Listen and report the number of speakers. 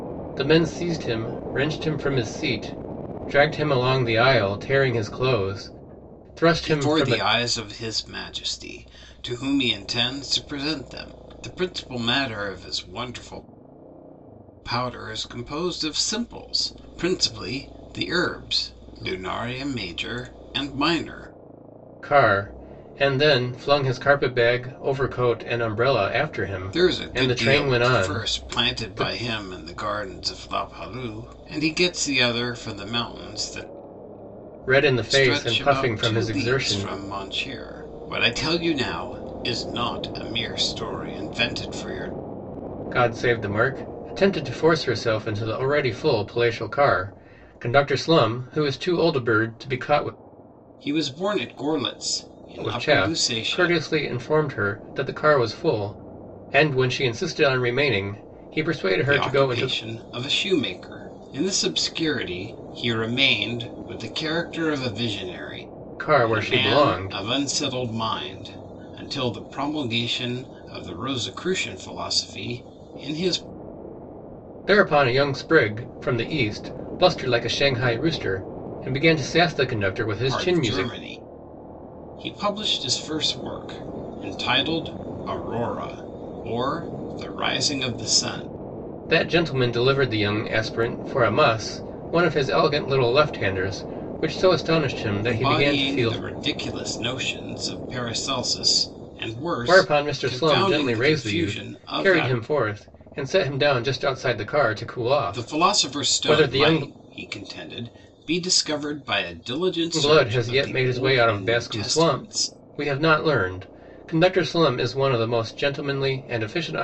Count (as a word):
two